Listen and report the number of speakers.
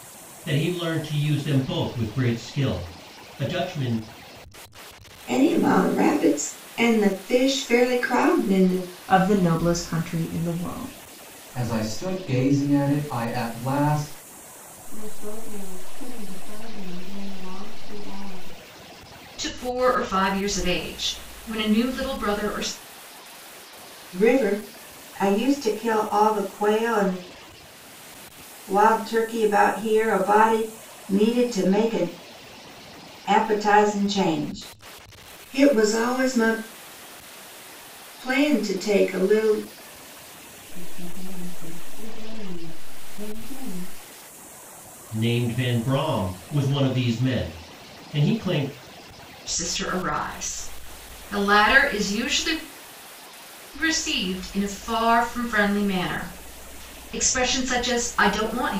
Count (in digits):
6